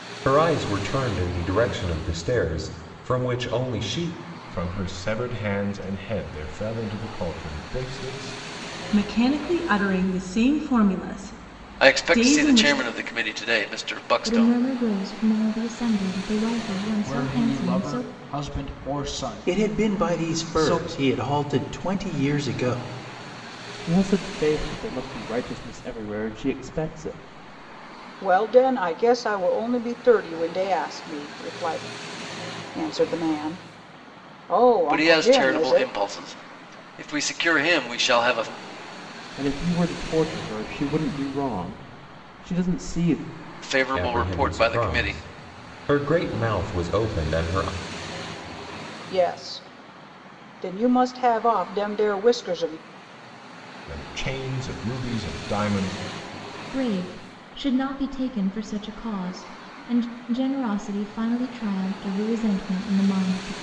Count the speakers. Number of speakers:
9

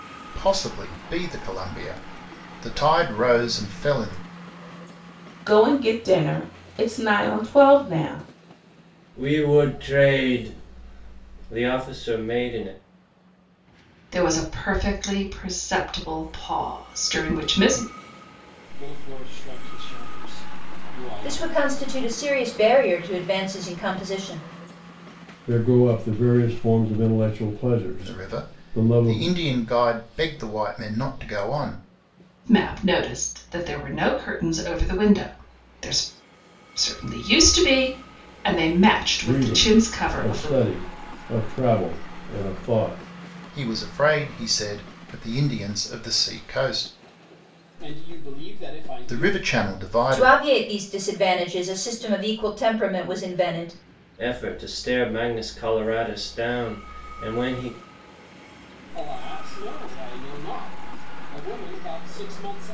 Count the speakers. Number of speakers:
7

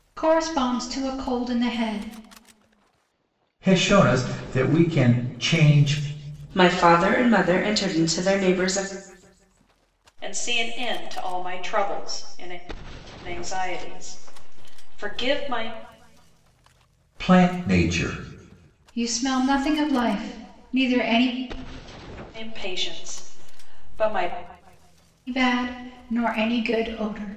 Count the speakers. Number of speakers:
4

